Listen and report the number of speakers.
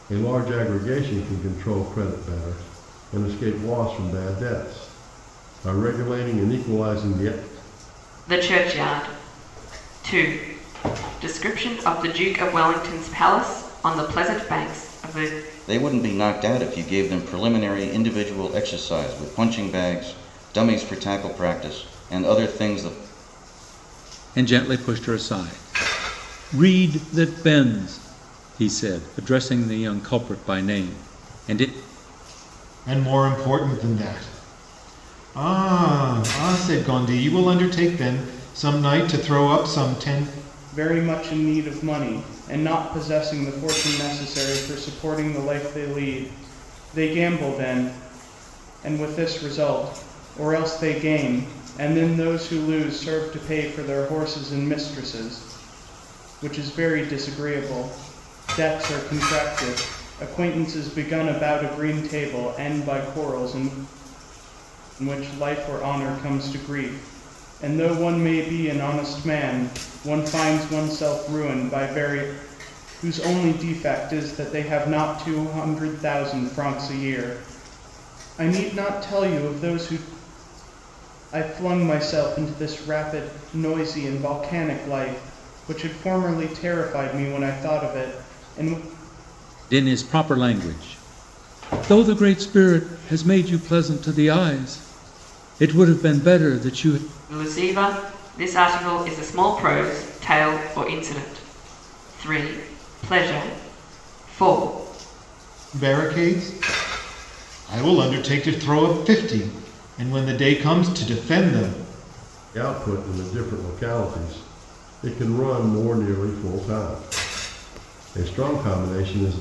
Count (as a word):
six